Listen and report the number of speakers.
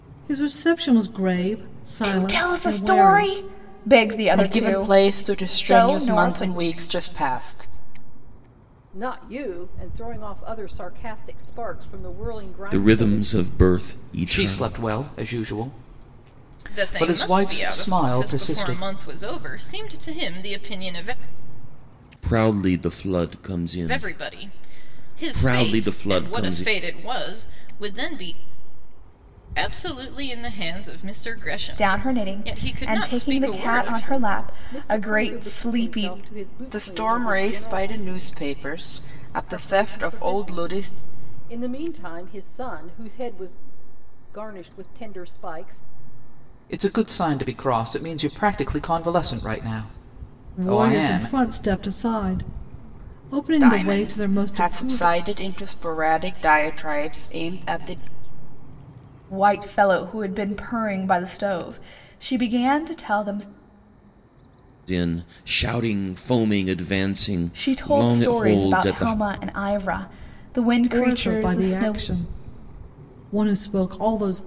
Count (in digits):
7